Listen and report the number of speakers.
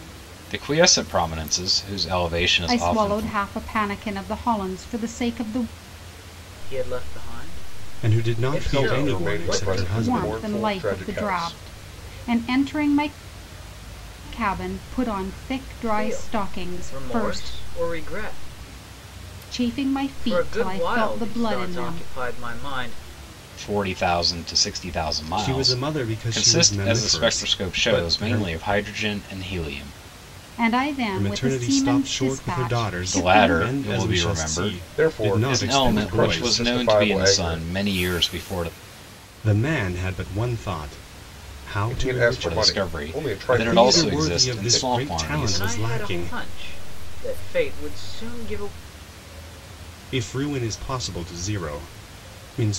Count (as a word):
five